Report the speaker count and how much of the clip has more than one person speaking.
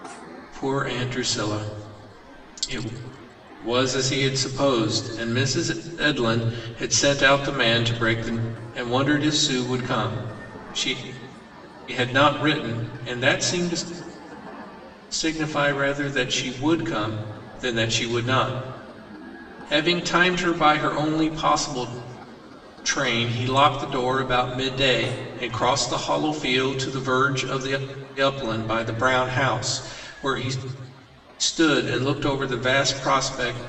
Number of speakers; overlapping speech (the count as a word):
one, no overlap